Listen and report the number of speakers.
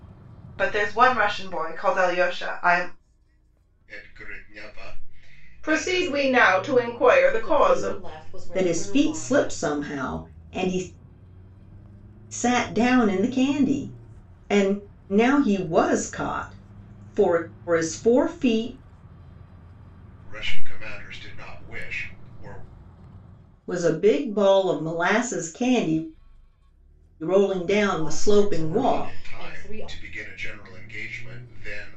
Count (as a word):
five